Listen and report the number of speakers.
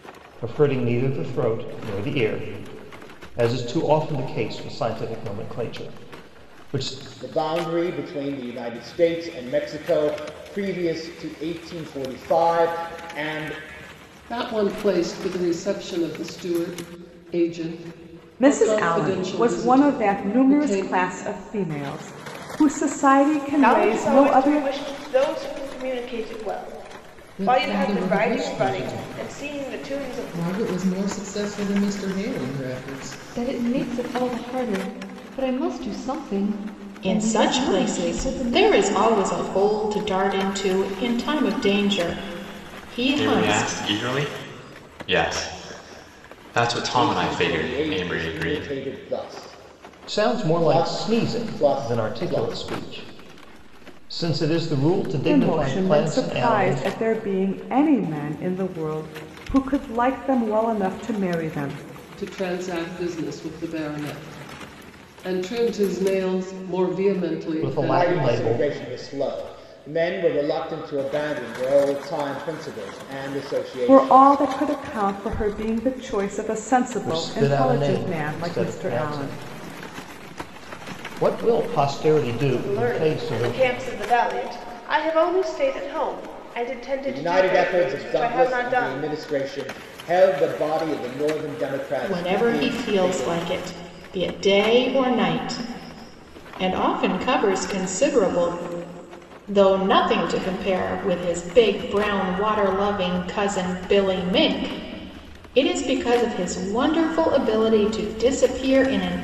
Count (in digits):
9